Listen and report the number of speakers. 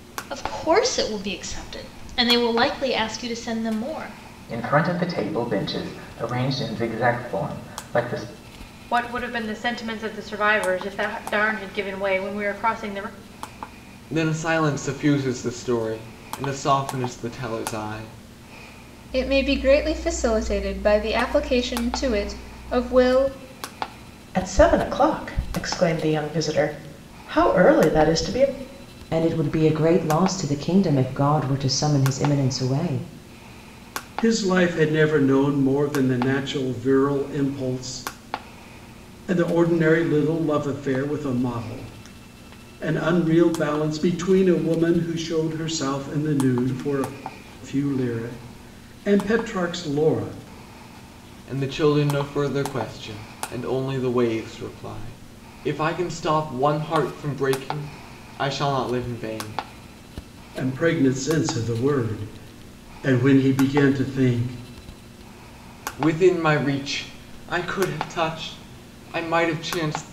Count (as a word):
eight